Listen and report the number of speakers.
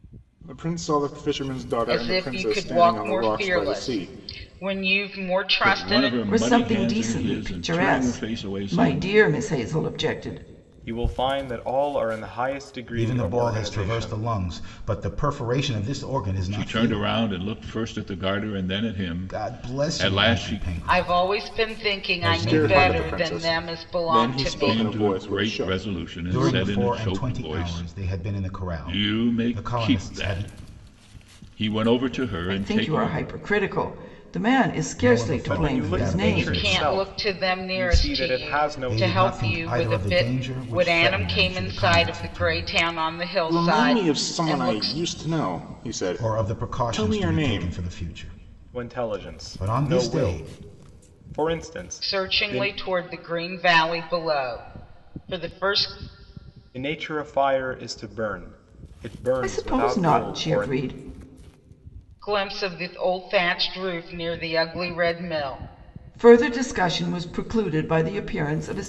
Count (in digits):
6